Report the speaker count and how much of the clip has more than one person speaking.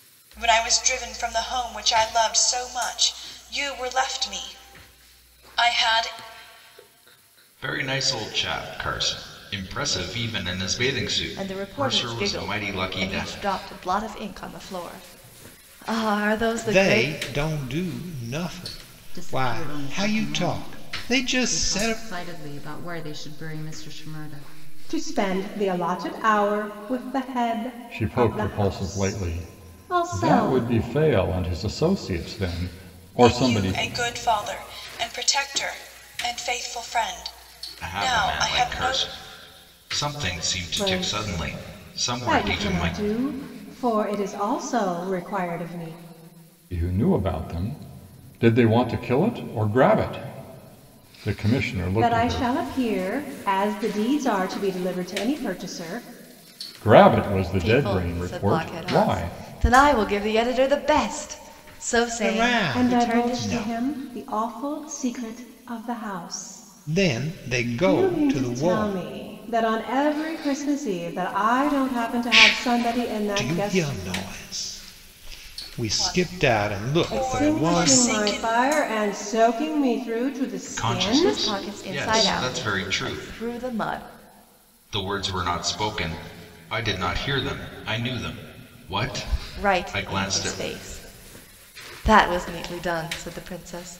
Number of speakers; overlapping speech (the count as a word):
seven, about 28%